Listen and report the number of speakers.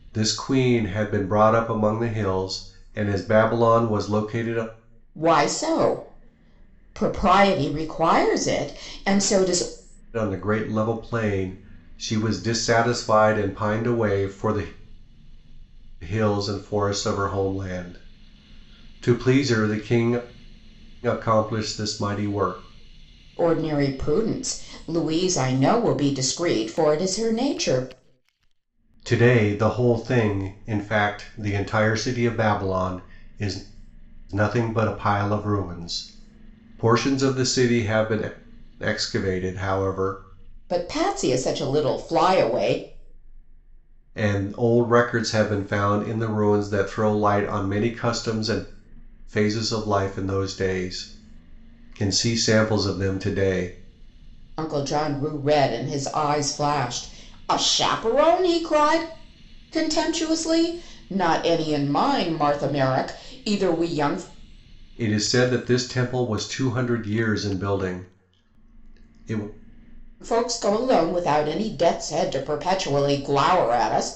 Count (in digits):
2